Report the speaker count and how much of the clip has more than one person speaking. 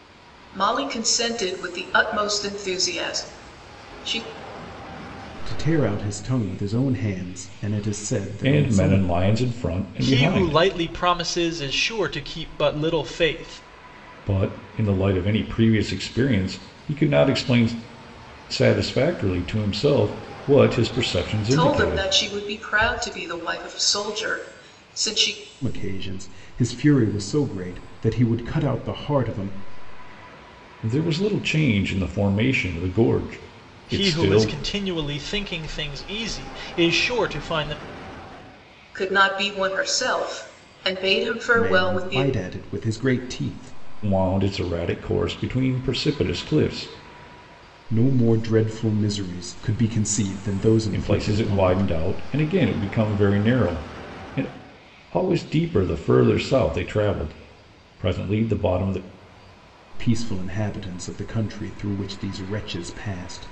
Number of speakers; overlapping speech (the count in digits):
4, about 7%